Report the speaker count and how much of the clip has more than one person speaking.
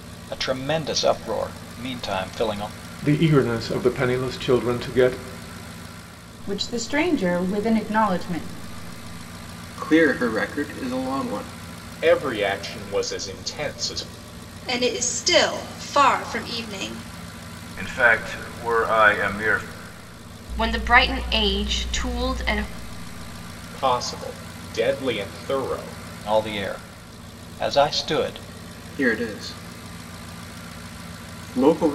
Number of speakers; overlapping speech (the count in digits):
8, no overlap